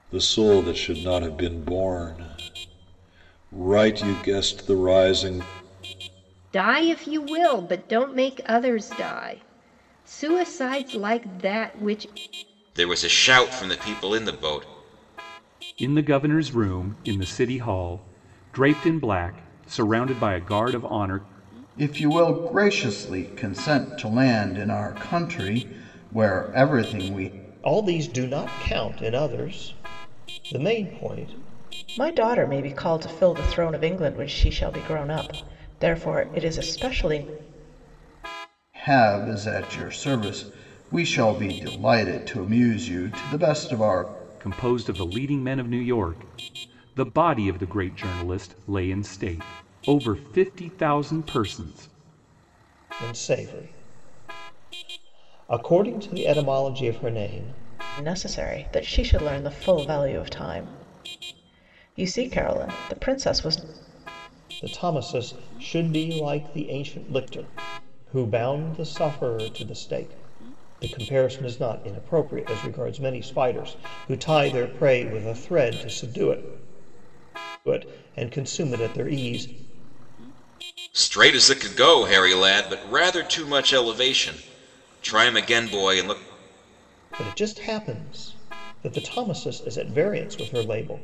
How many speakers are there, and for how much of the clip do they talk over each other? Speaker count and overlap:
seven, no overlap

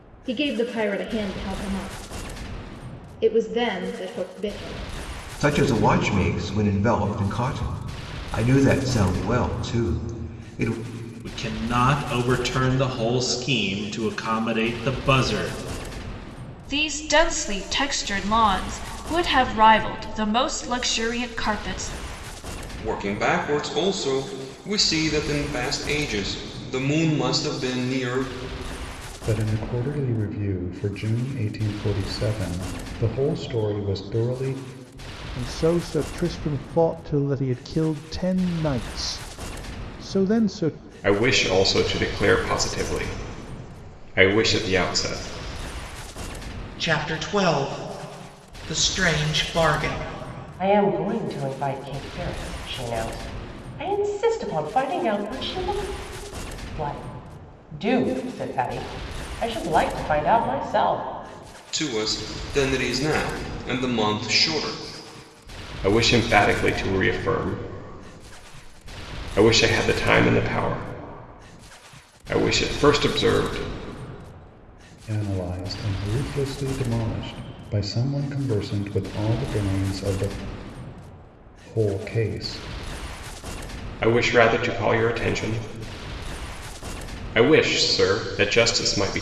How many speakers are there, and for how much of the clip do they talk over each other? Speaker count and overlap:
ten, no overlap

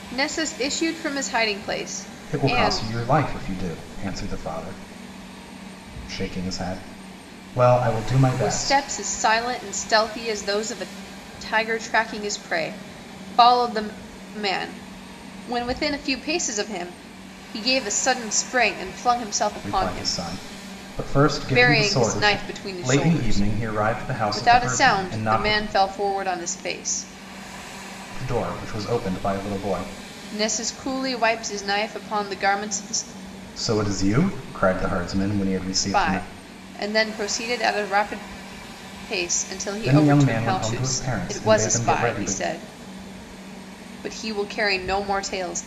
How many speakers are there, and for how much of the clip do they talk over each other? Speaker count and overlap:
two, about 17%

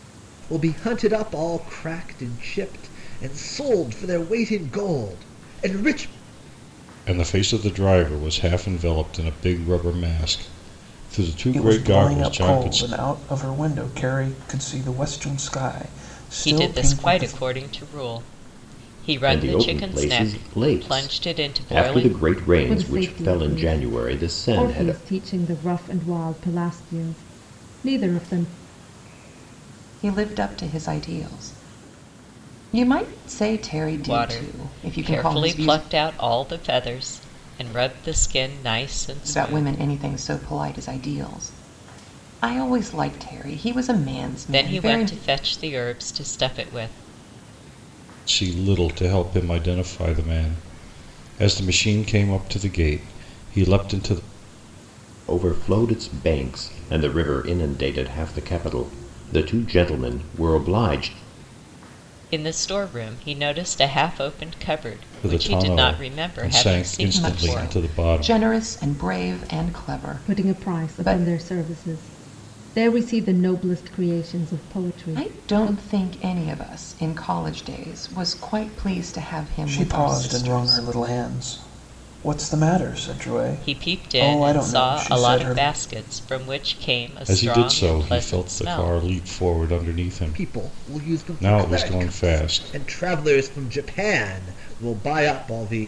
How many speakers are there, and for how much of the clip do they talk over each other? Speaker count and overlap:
seven, about 24%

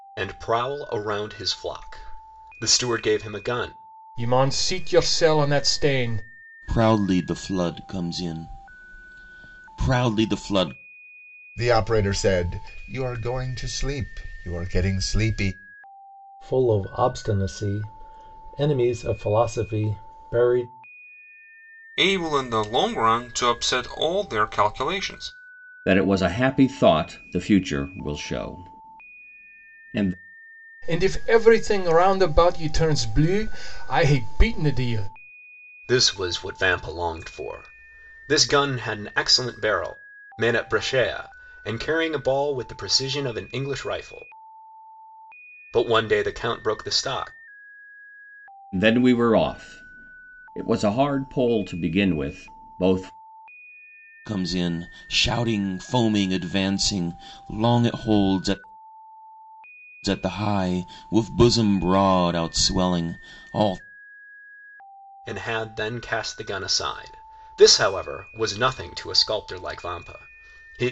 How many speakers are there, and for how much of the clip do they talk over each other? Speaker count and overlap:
seven, no overlap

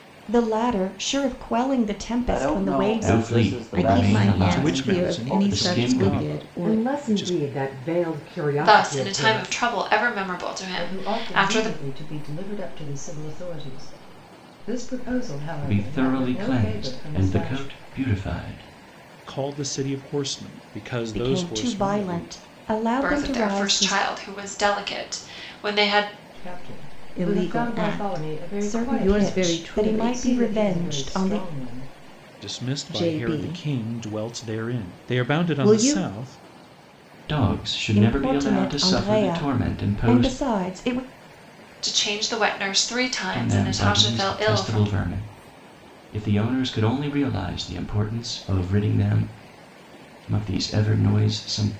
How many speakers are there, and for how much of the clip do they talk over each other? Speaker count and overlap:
eight, about 45%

